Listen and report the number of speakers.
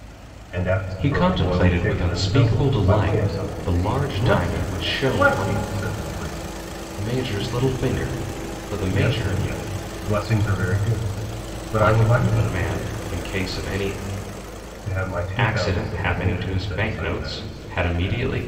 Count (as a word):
two